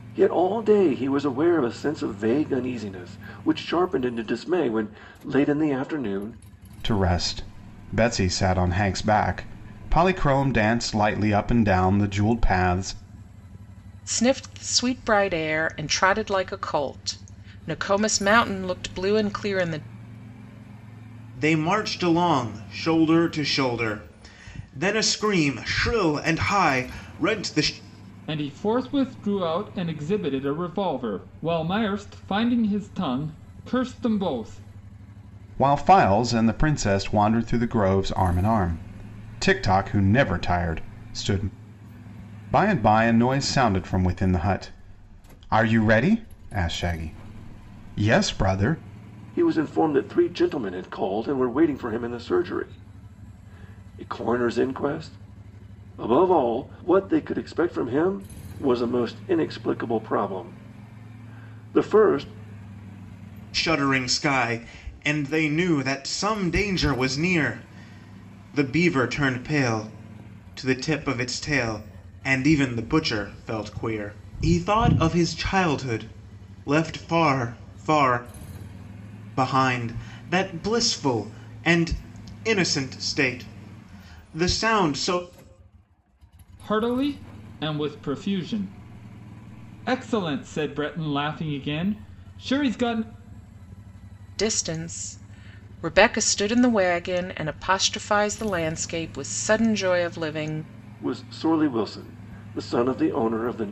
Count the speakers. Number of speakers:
5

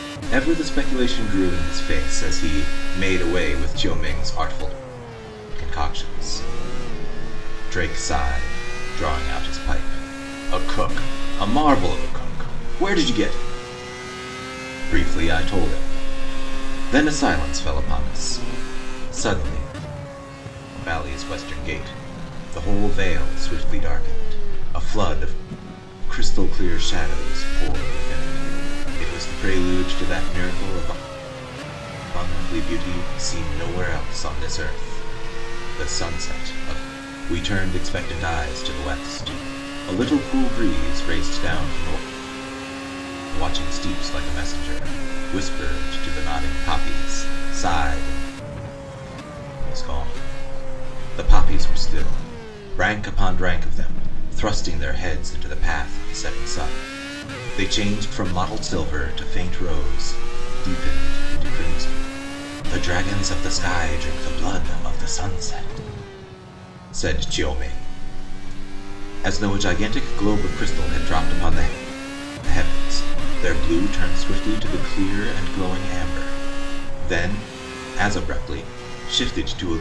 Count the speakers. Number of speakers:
1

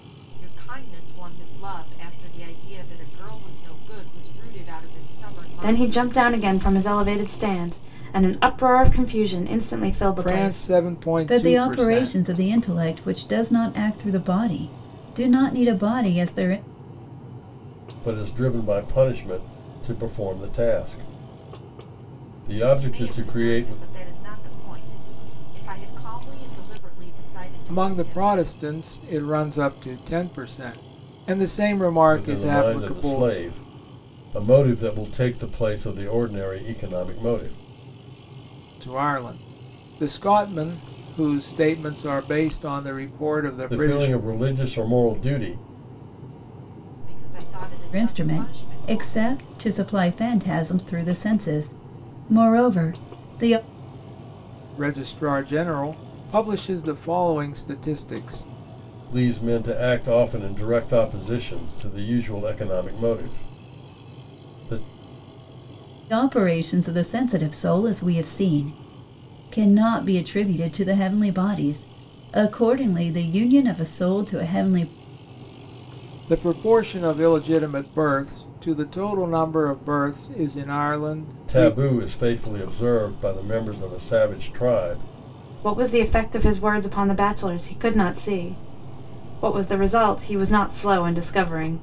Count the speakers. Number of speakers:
5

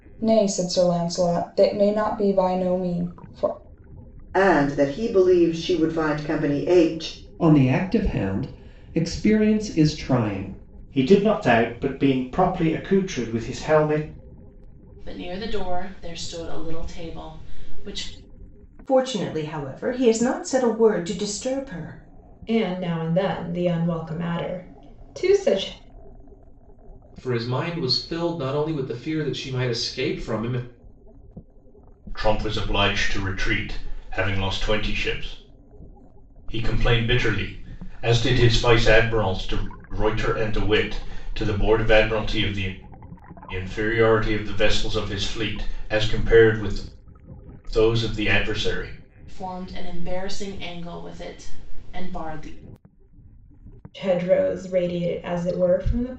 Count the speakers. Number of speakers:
9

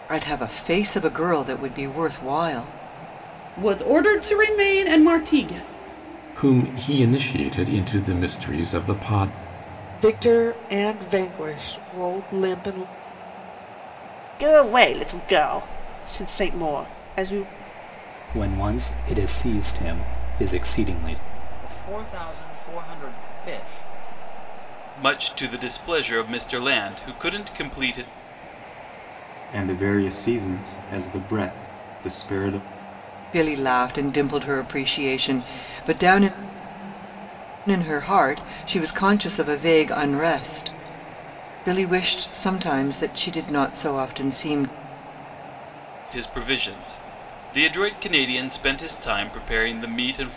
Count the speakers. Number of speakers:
9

